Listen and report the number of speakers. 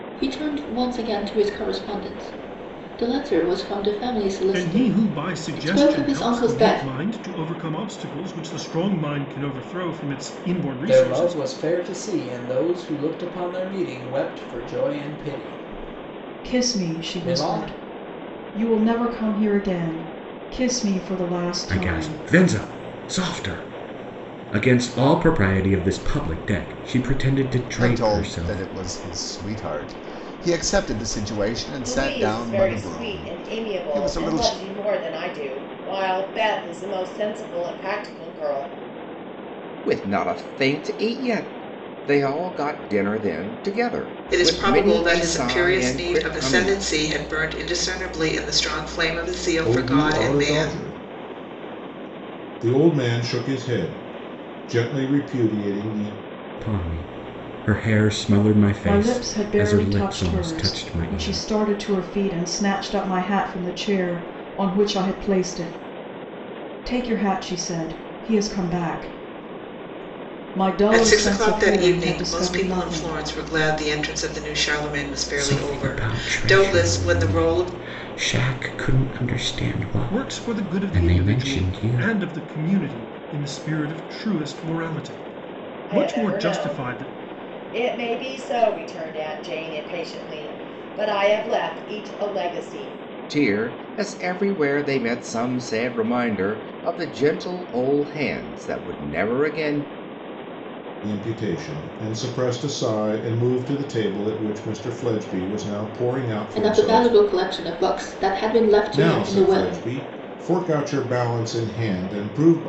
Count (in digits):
10